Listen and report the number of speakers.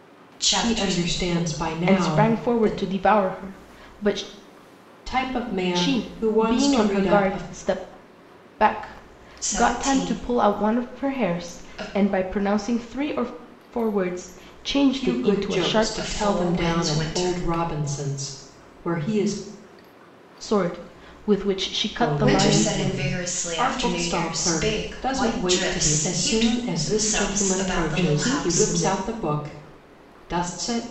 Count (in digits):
3